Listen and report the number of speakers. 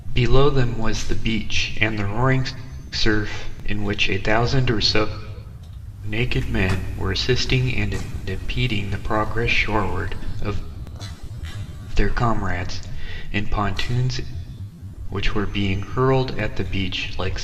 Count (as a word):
one